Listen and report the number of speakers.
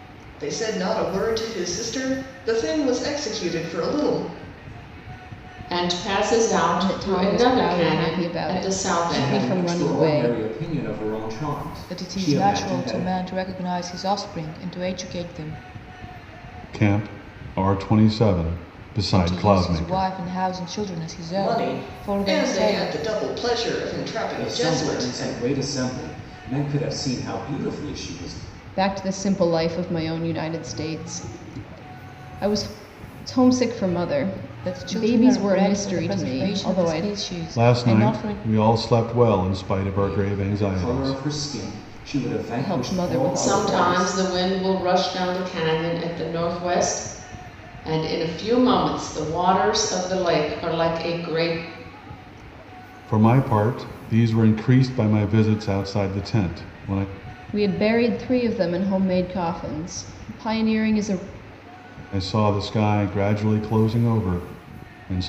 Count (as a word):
six